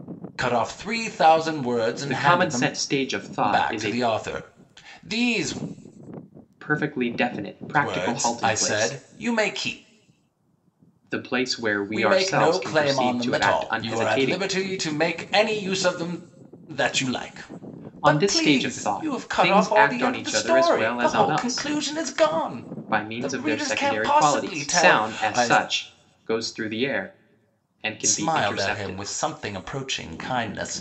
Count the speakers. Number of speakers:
2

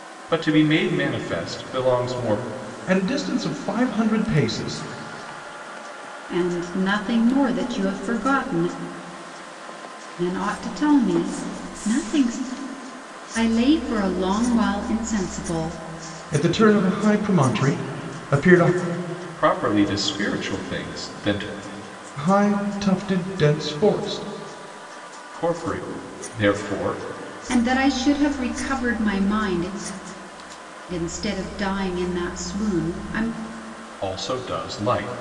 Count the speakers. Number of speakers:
3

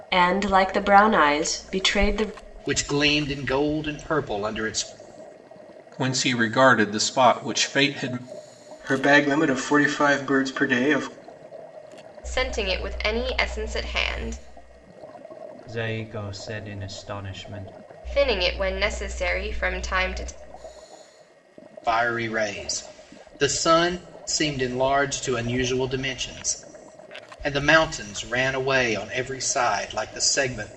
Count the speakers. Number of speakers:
6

